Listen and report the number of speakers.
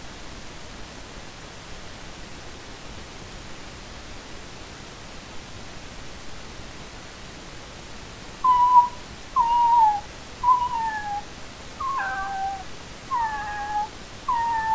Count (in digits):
0